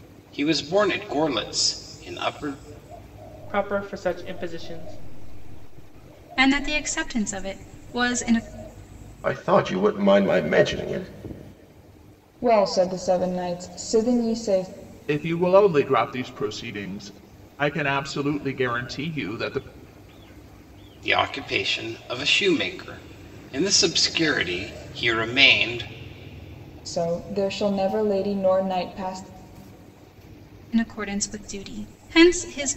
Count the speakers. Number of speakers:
6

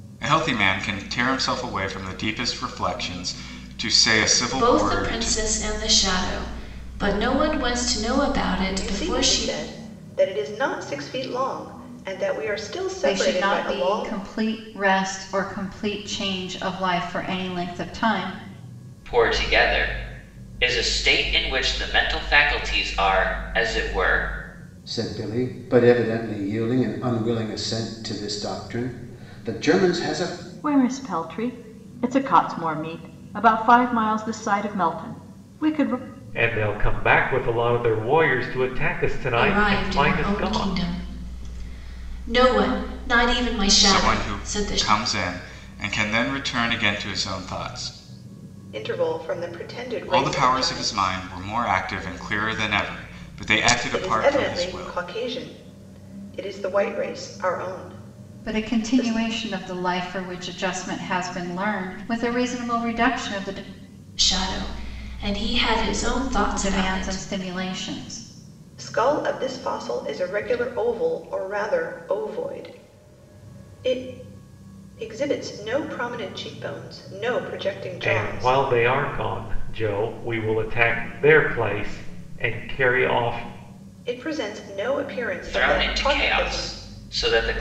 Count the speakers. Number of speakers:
8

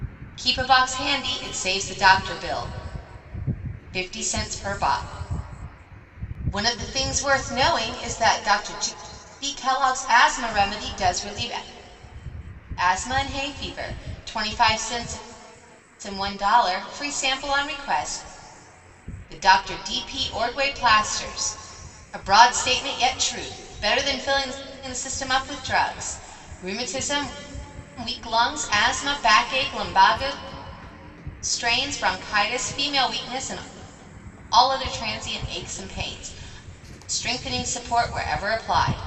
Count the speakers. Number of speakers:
1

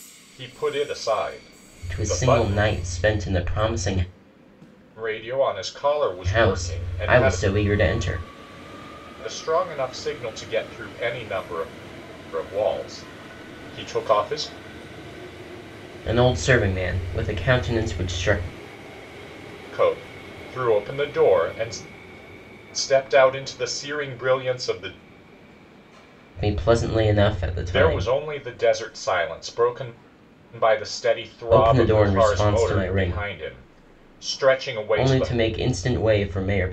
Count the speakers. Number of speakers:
2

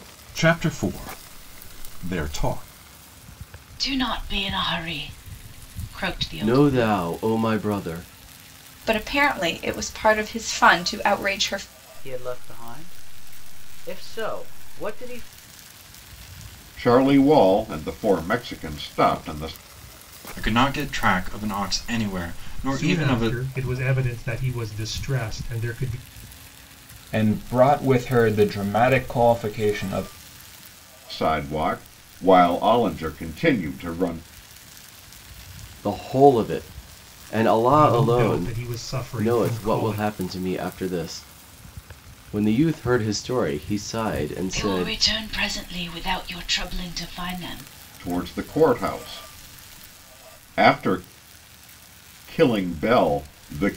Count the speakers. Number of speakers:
9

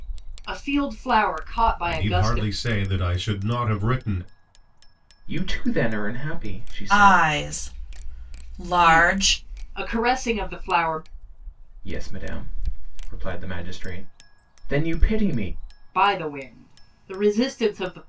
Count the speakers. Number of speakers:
4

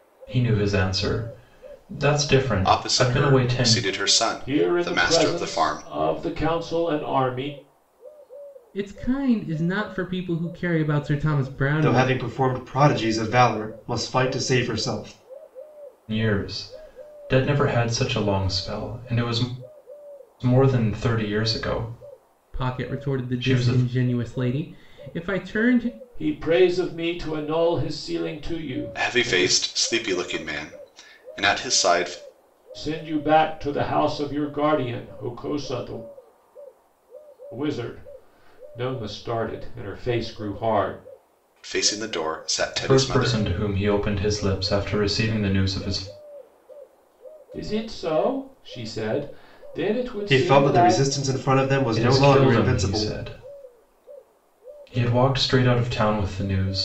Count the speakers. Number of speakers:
5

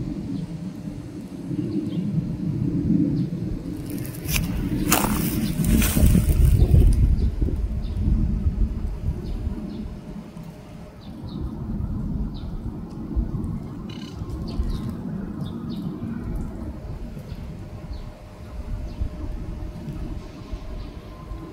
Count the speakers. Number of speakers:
0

